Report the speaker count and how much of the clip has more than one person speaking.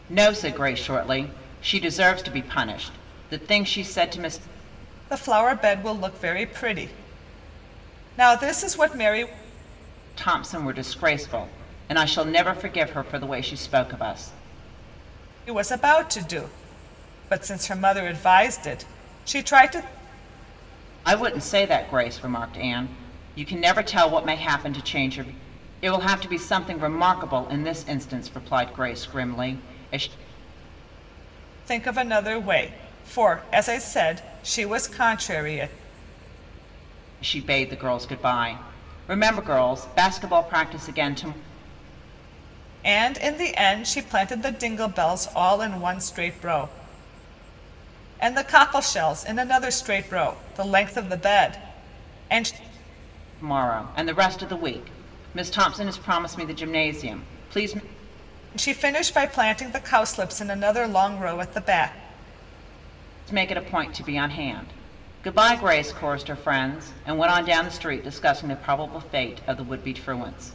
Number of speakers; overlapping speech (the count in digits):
2, no overlap